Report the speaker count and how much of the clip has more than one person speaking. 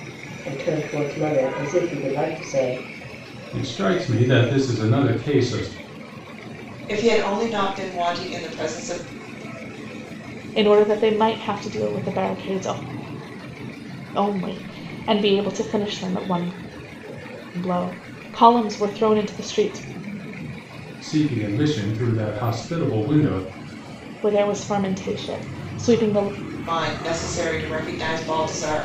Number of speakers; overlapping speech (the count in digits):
4, no overlap